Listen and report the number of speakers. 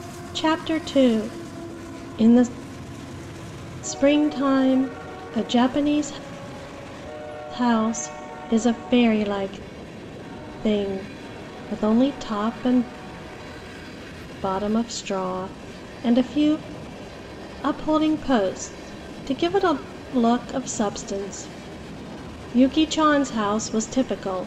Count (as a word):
one